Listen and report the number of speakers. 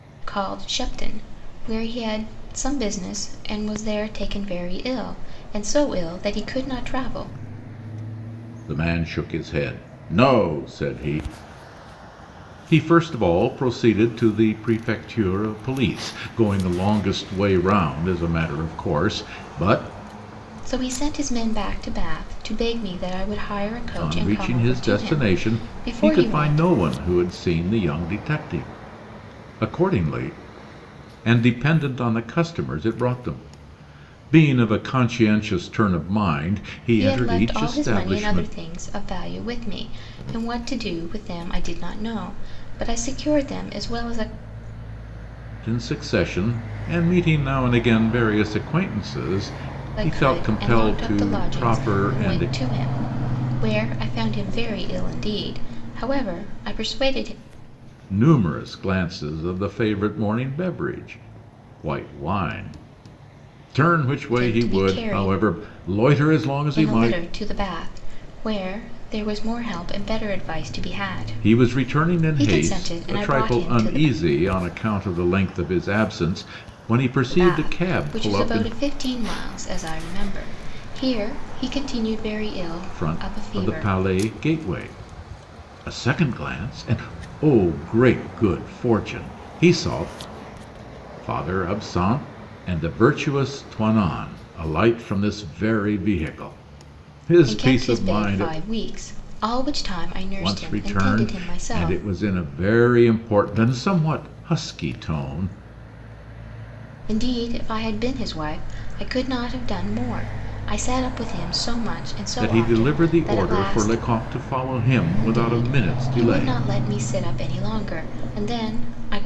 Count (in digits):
2